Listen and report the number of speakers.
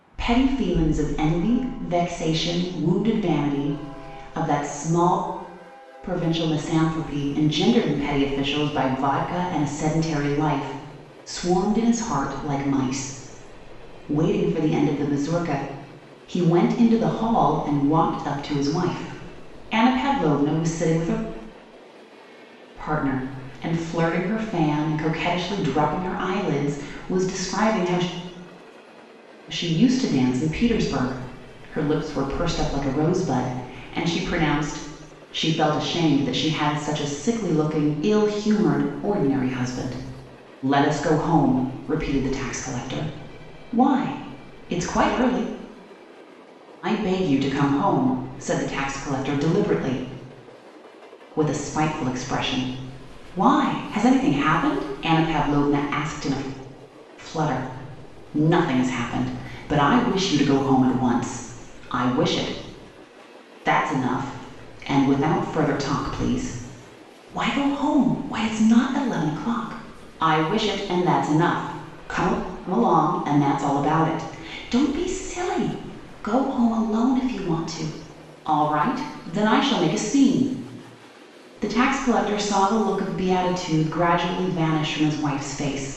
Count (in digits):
1